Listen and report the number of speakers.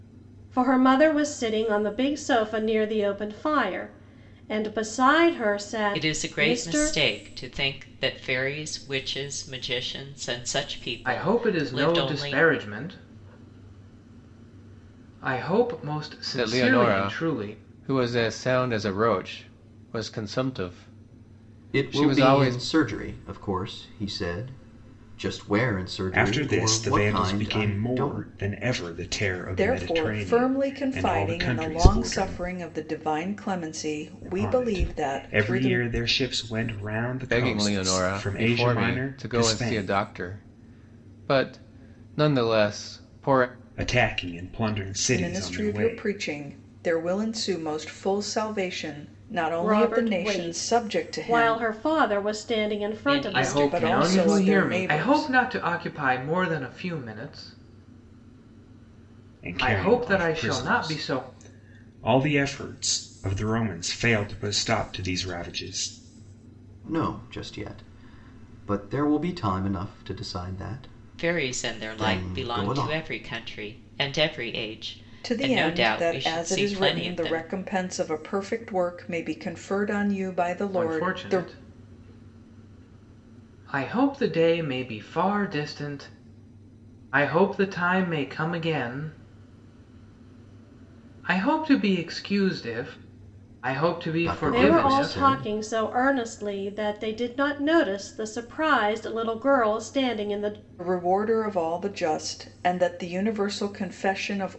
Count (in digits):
7